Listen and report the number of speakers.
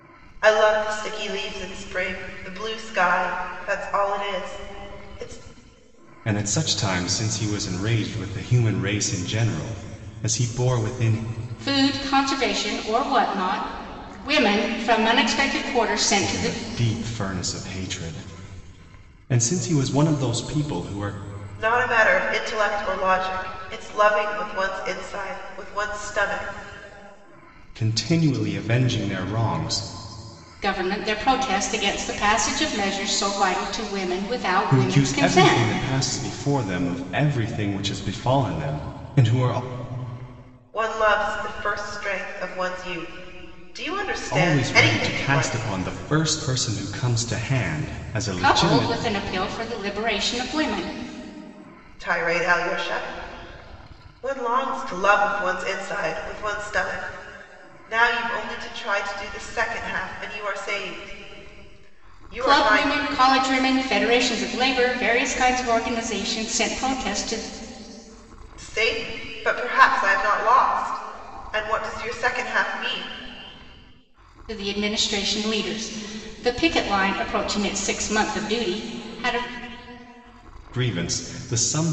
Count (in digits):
3